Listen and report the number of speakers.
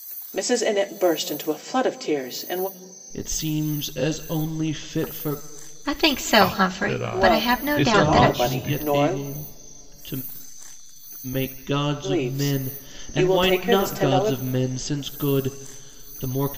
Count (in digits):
4